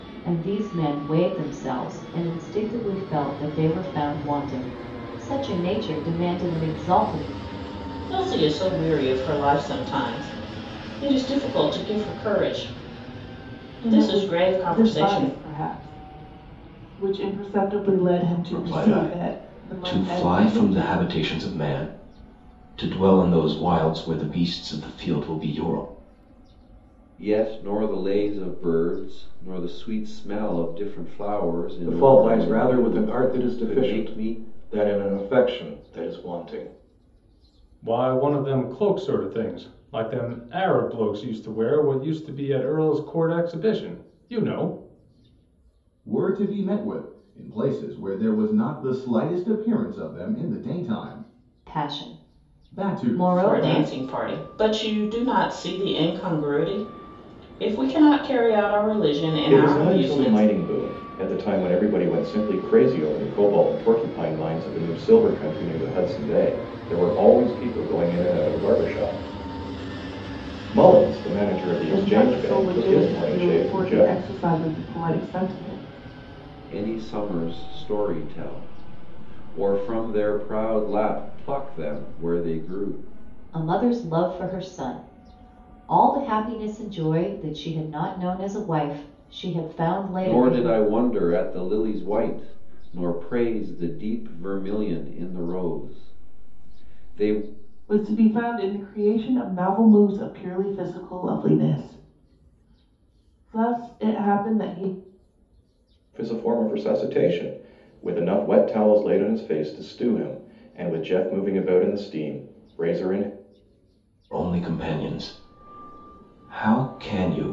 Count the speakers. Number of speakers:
8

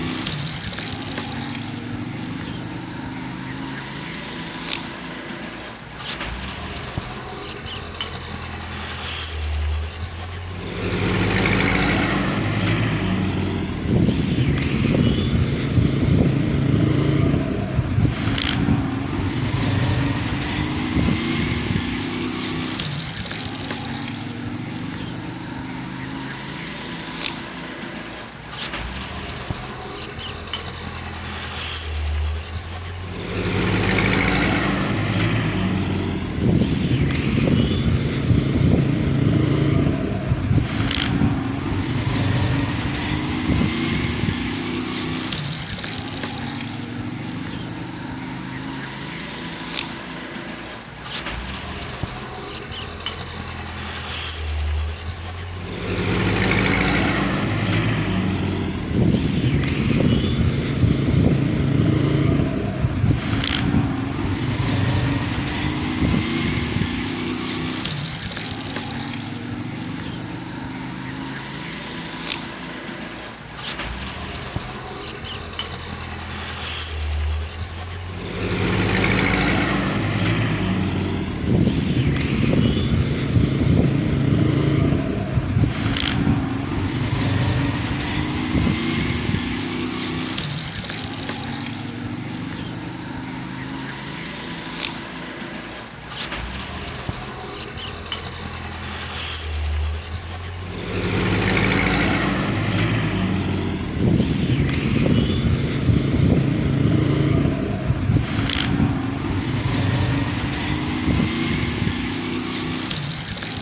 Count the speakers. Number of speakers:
0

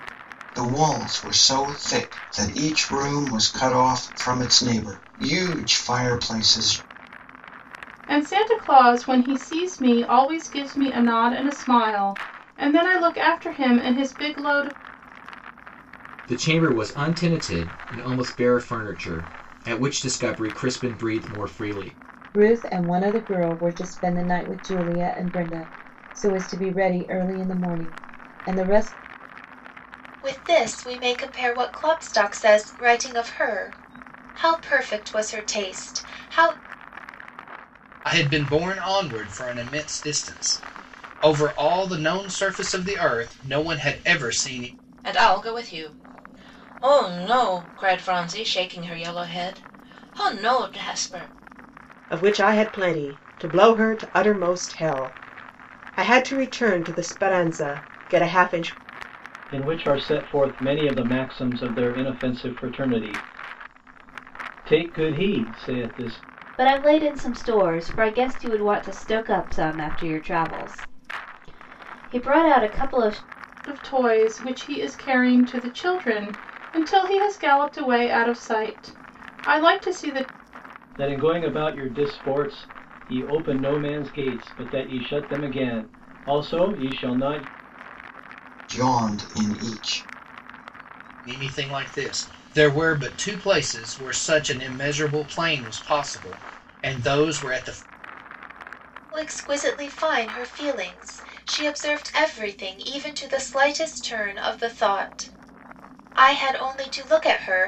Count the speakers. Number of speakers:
10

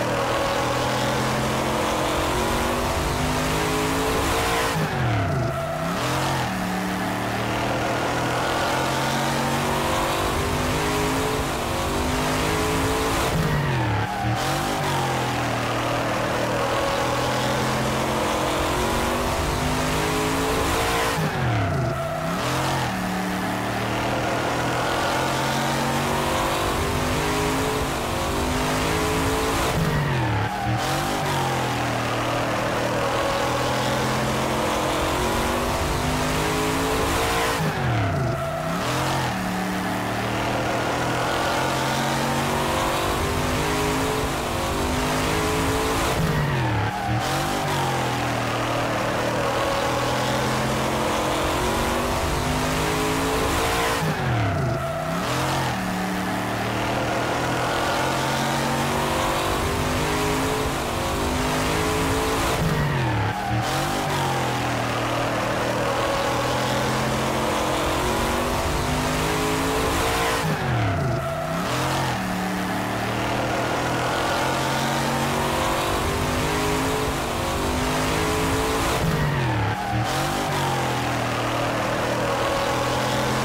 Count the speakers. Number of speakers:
0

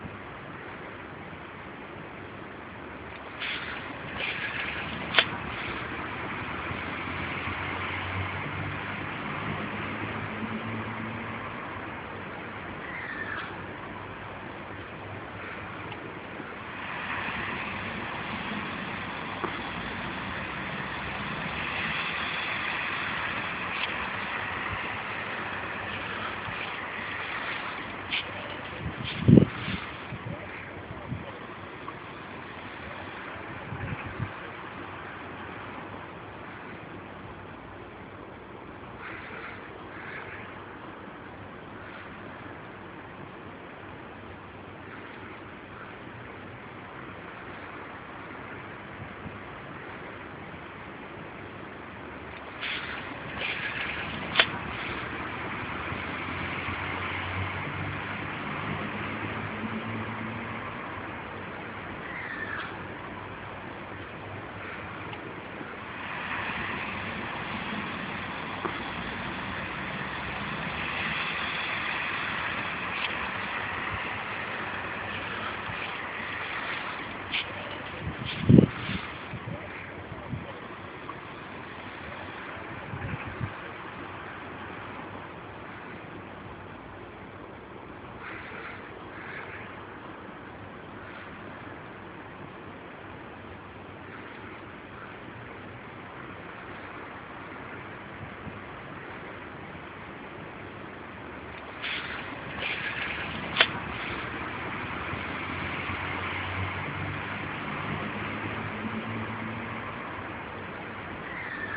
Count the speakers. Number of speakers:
0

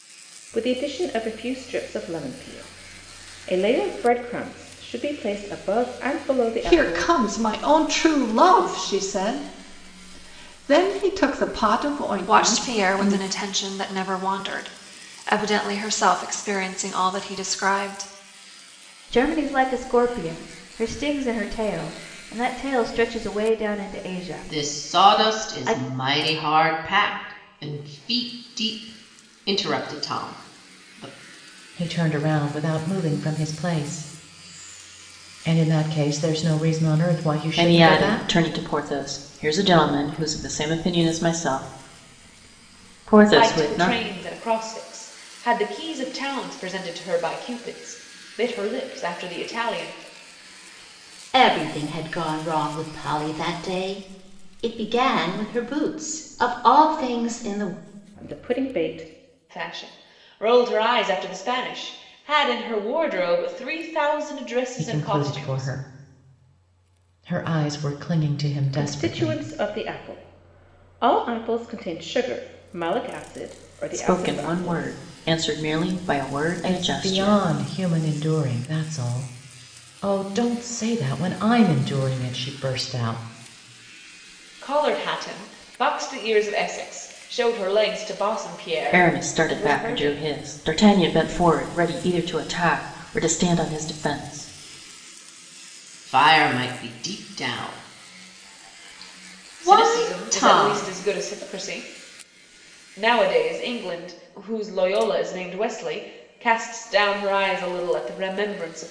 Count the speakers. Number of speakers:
9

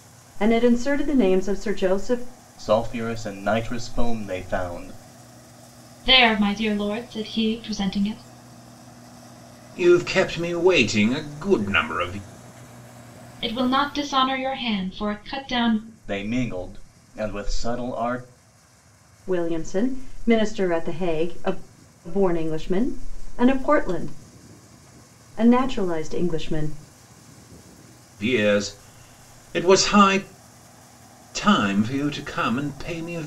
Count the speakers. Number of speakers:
4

